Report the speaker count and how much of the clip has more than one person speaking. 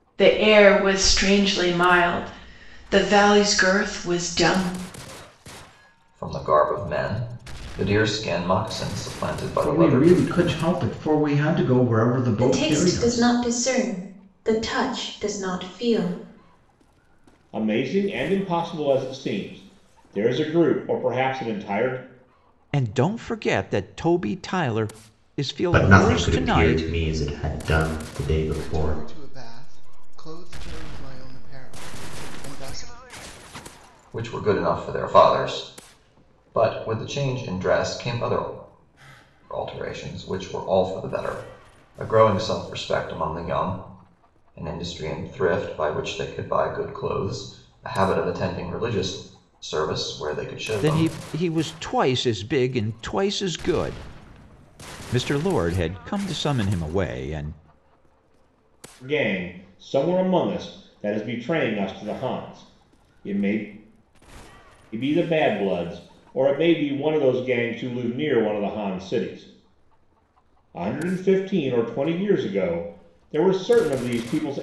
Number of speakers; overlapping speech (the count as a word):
eight, about 5%